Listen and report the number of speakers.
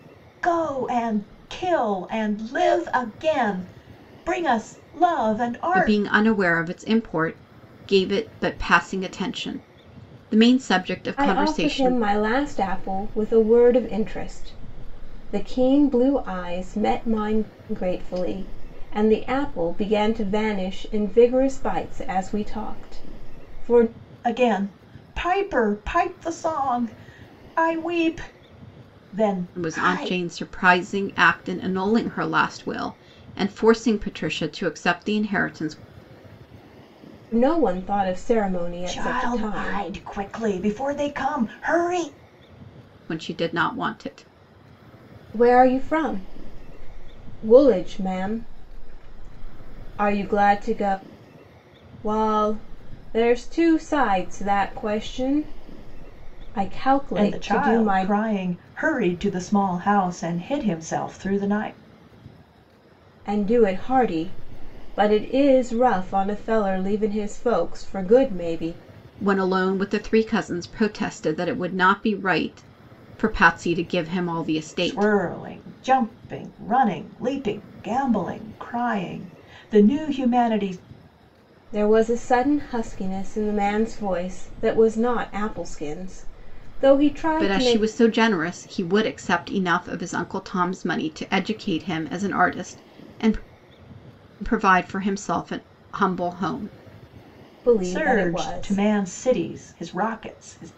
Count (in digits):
3